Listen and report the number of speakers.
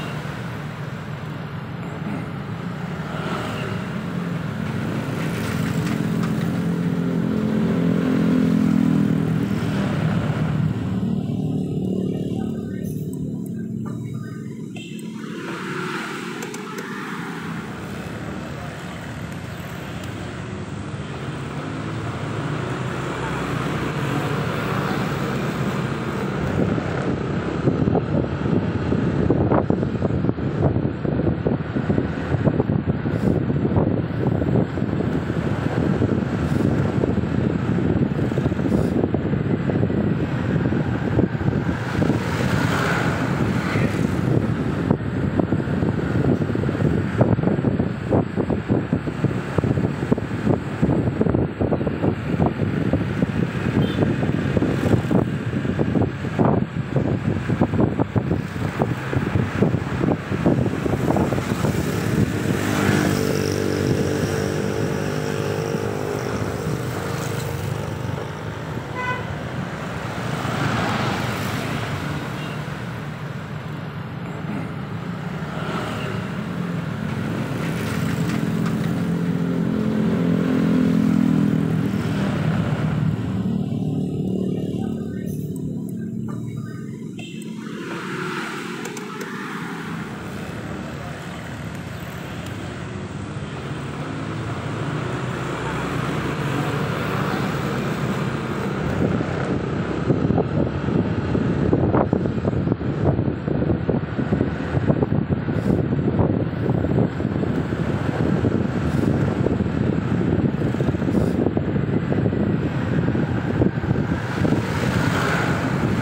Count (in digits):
0